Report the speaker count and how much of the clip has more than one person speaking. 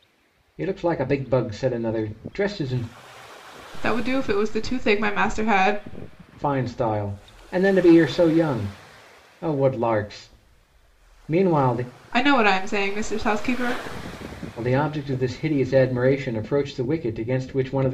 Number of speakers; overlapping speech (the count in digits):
2, no overlap